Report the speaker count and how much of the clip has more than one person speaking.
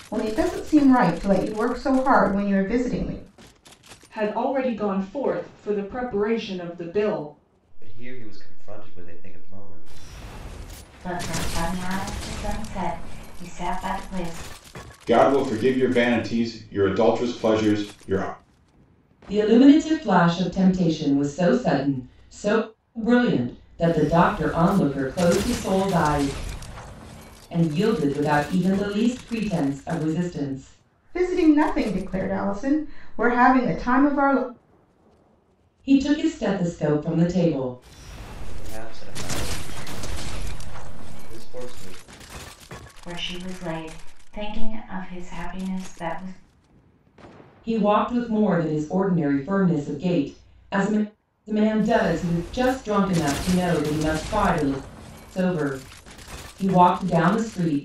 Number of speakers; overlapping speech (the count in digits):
6, no overlap